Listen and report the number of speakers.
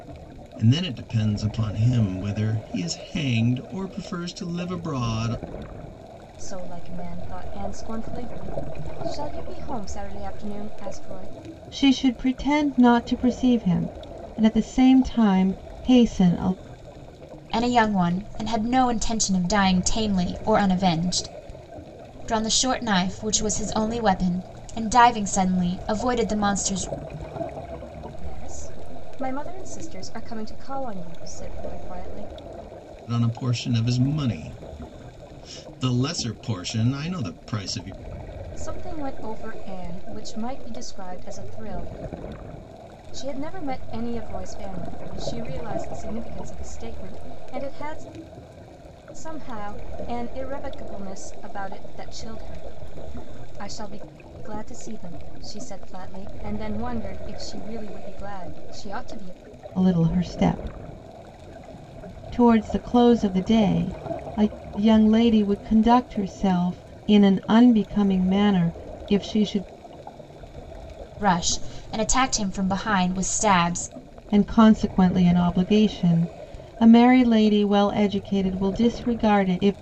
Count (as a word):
four